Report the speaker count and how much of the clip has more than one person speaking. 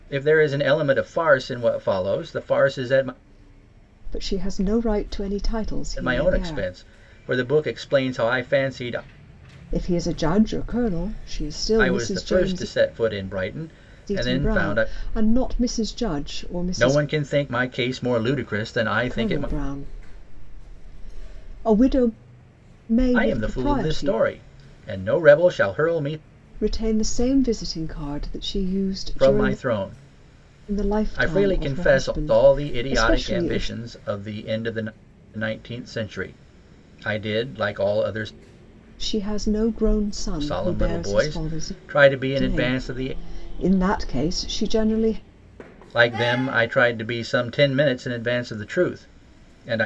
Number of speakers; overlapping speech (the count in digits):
2, about 19%